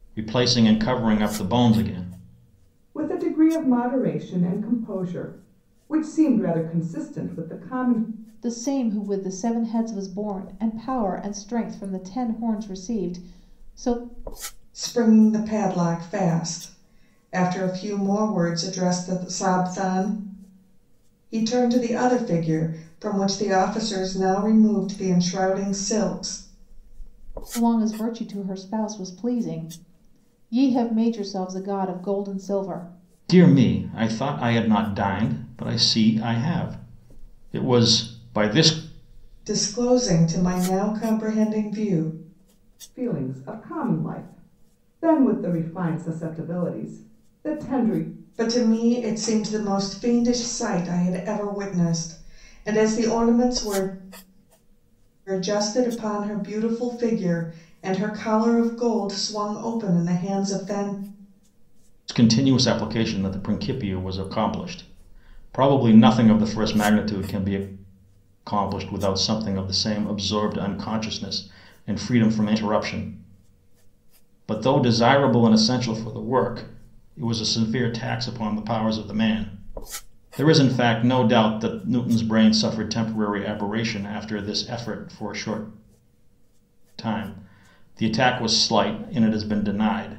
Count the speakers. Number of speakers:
4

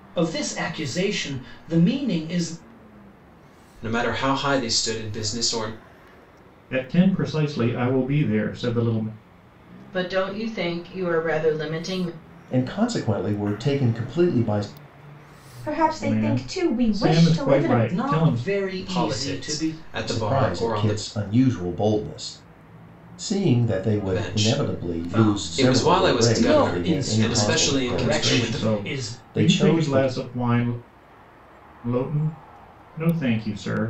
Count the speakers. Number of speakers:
6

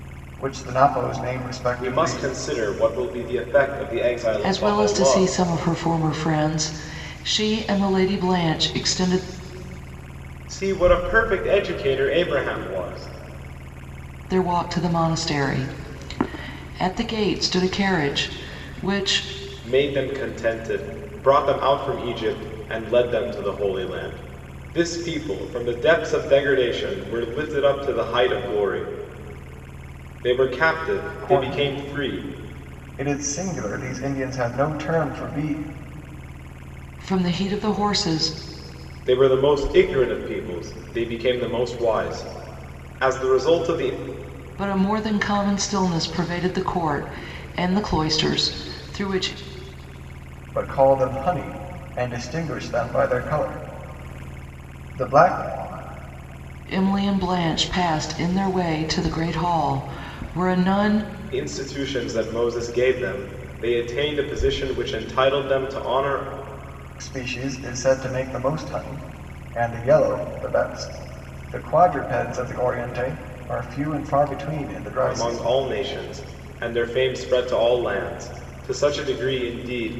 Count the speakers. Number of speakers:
3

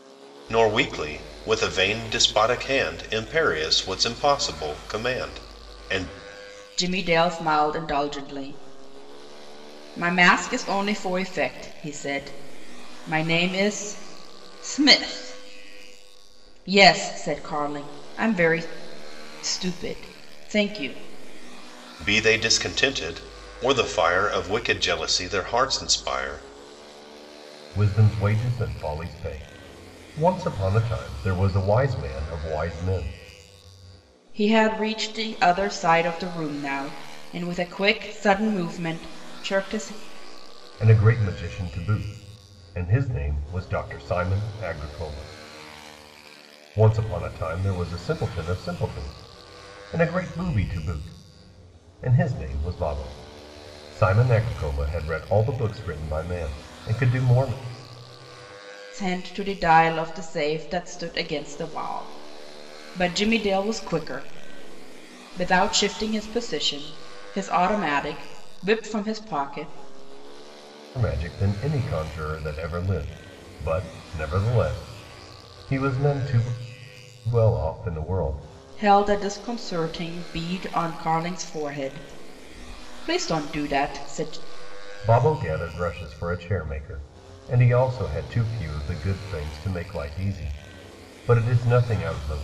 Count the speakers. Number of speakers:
2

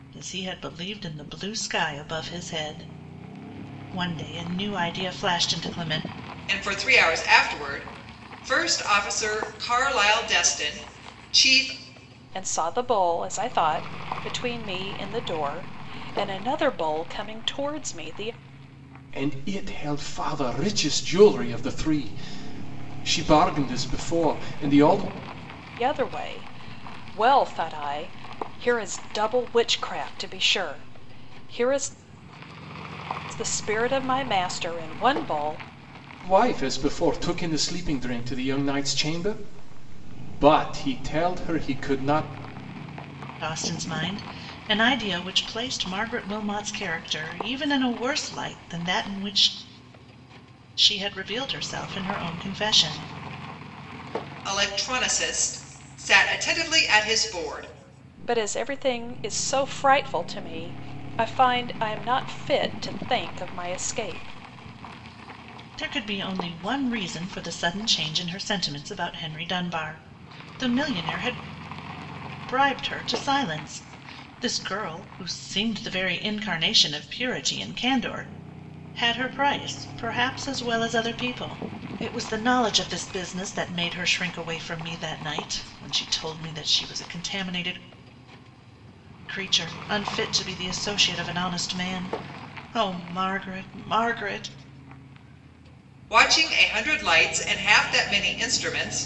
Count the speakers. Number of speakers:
4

